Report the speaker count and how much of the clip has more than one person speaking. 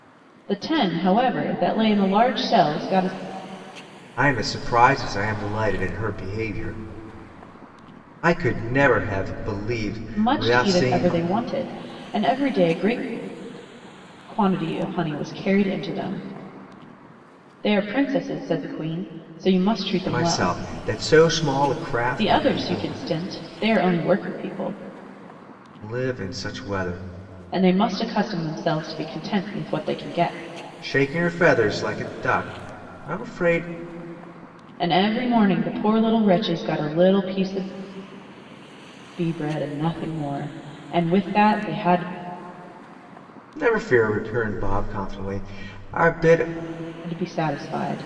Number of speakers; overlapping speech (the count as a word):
two, about 5%